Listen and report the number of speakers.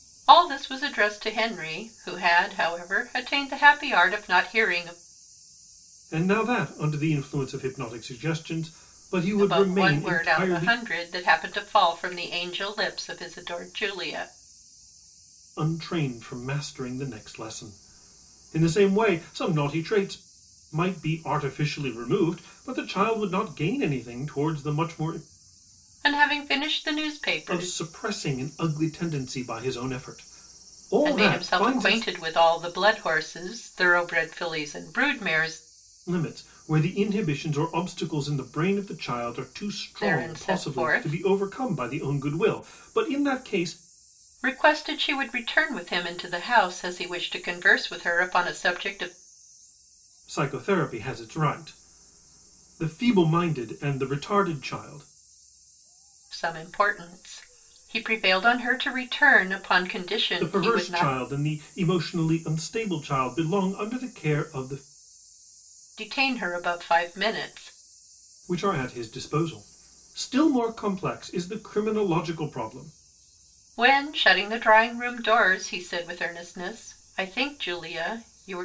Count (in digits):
2